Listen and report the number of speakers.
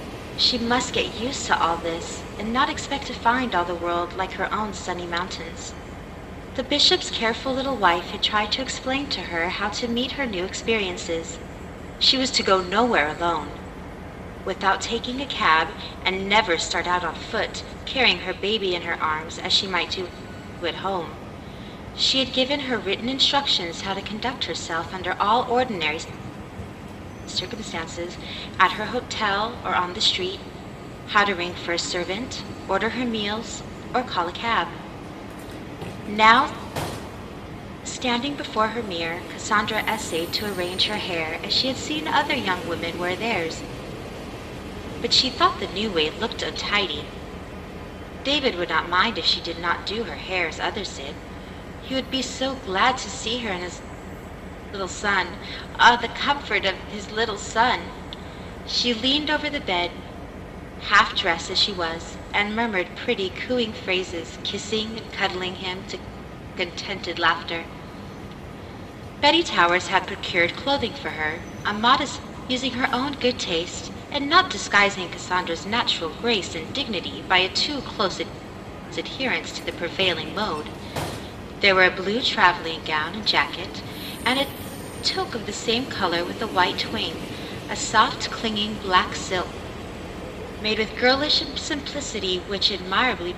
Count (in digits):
1